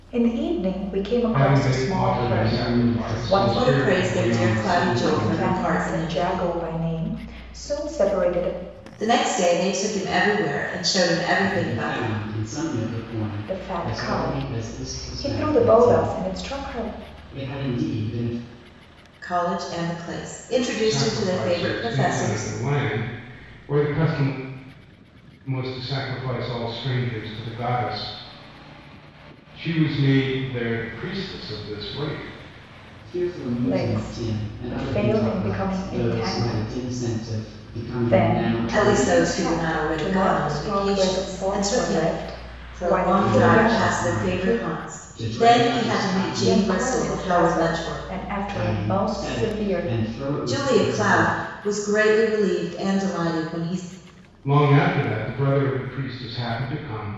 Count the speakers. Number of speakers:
four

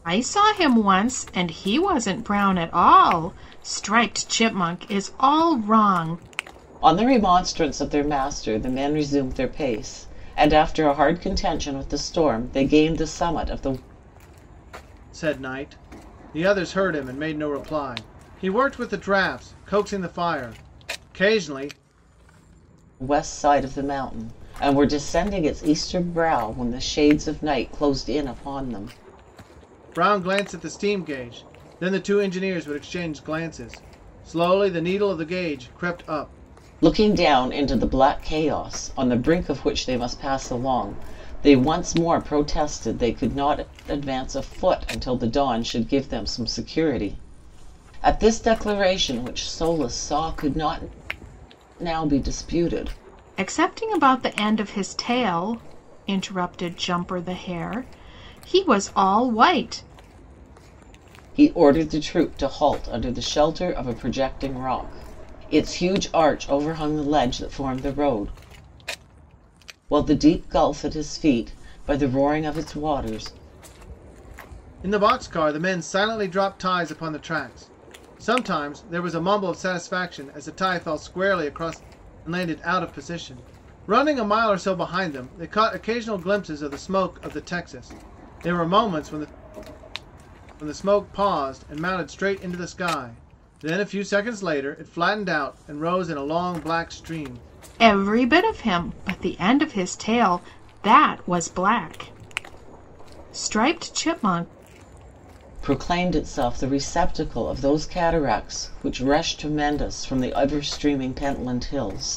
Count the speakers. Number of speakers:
three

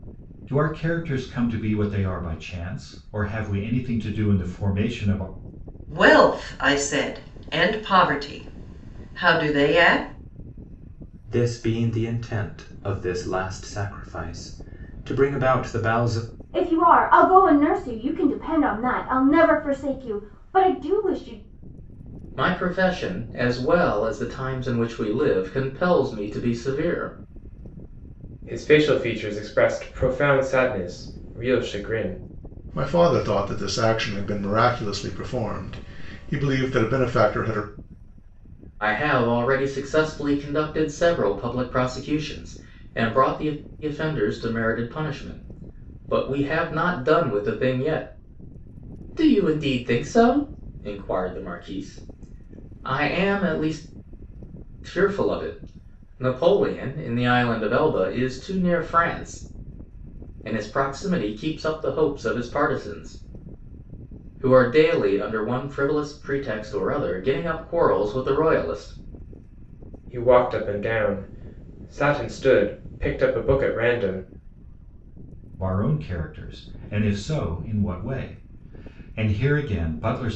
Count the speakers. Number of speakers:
seven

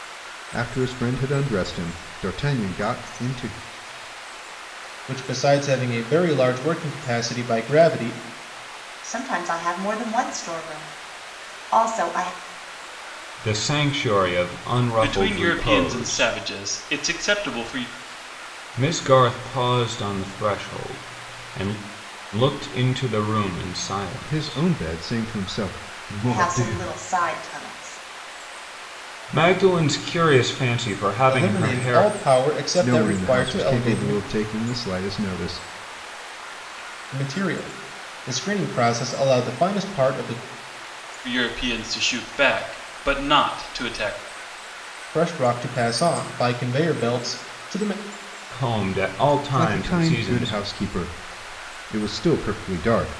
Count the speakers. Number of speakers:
five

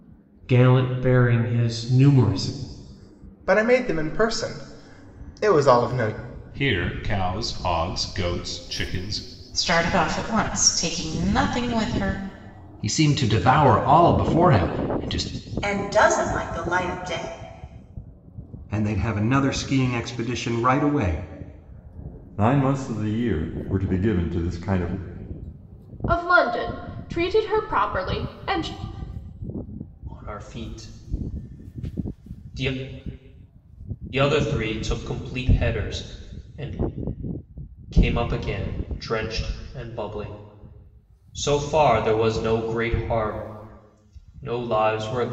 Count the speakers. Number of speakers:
ten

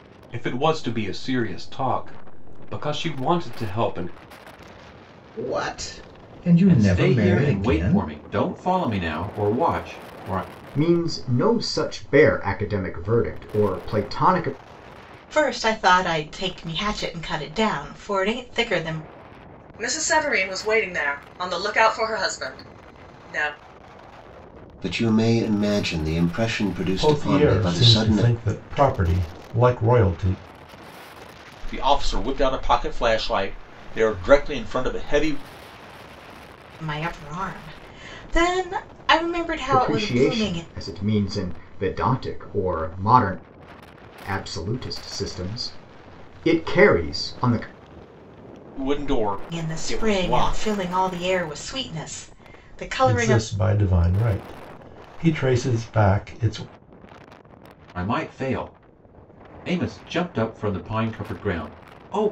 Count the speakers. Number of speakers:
nine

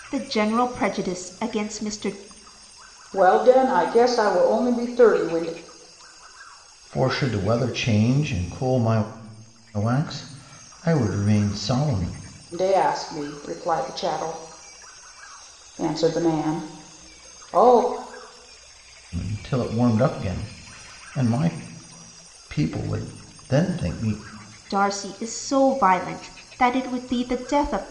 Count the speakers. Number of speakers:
three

